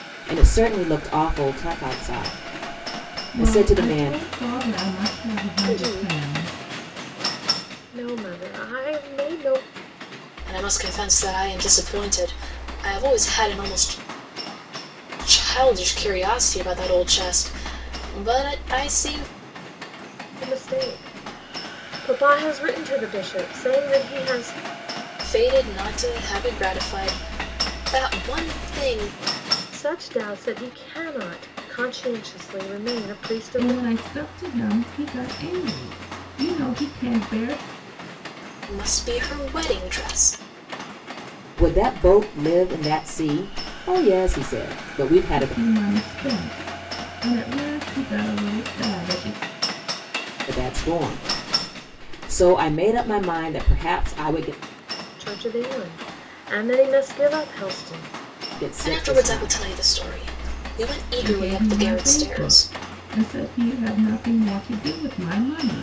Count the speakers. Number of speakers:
four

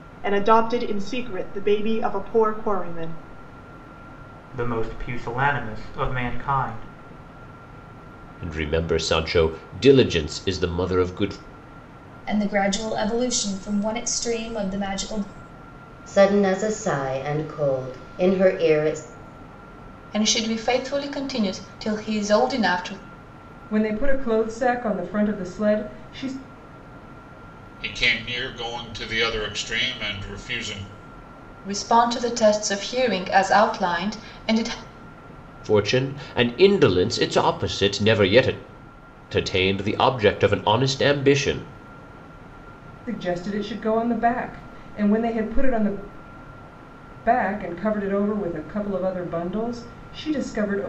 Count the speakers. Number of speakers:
eight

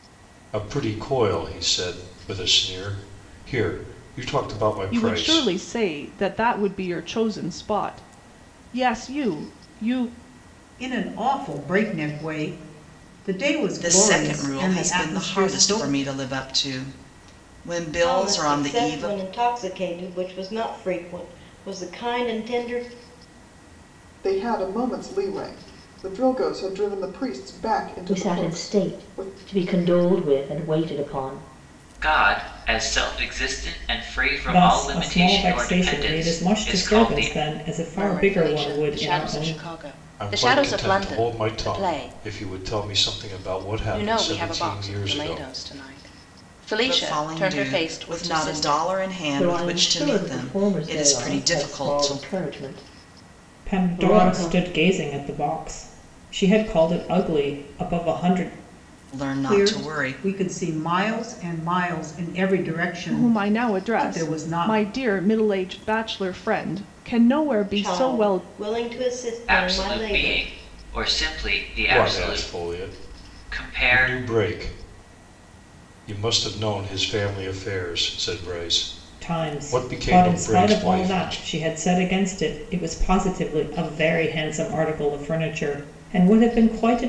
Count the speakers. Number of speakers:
ten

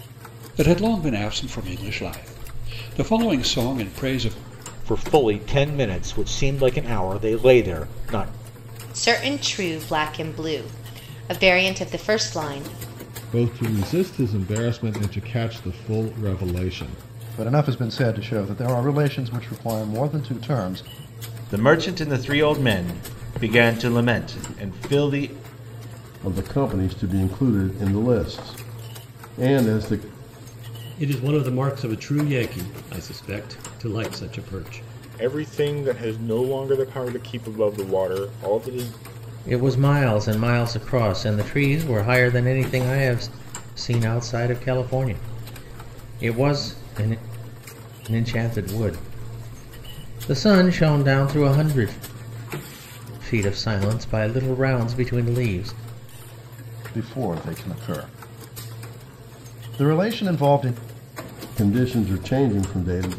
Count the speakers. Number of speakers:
ten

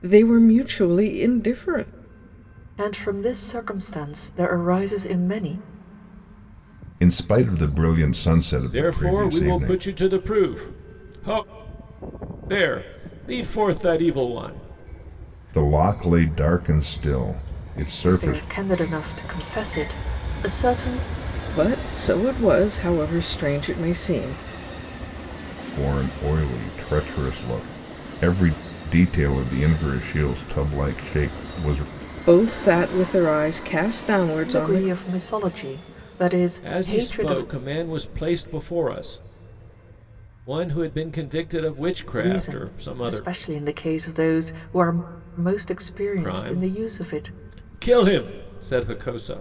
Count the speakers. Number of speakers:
four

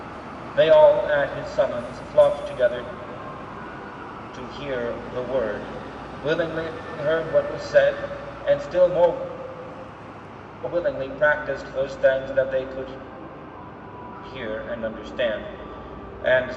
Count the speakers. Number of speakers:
one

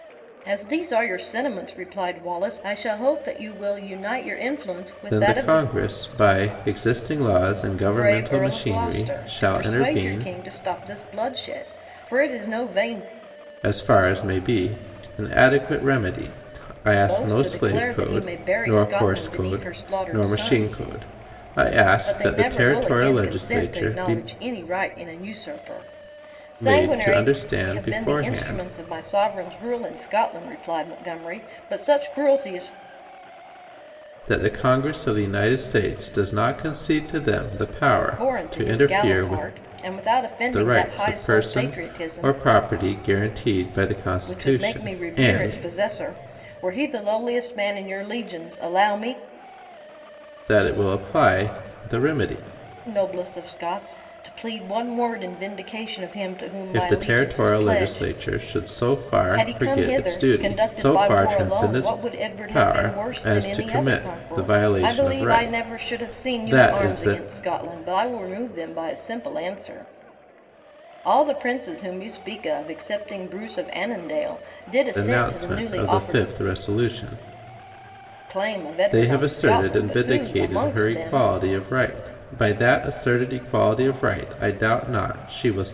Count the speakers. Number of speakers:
two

